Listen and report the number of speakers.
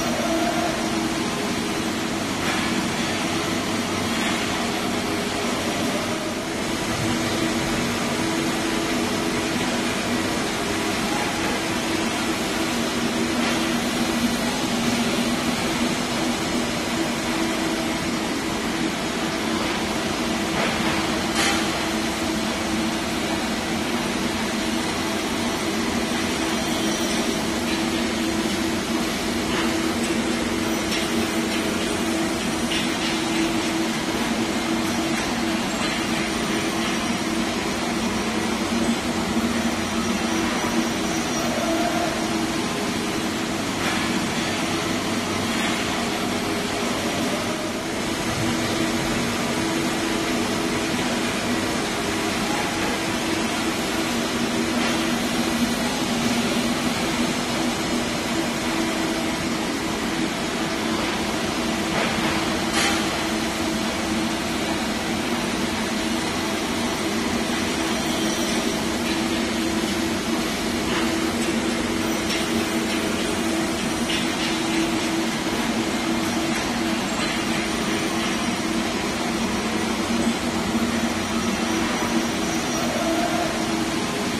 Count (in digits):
0